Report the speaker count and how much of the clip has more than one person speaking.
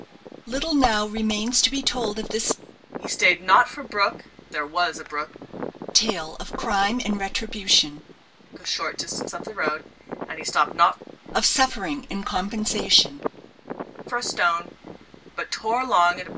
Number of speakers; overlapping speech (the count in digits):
2, no overlap